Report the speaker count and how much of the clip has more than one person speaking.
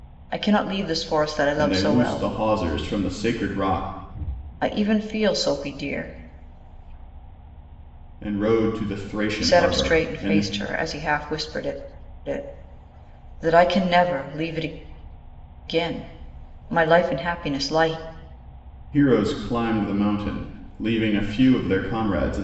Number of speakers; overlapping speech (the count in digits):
2, about 8%